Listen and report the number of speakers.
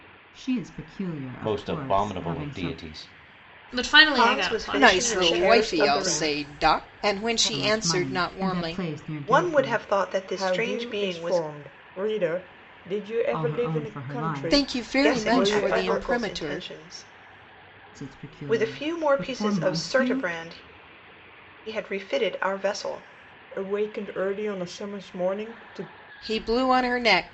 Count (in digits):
6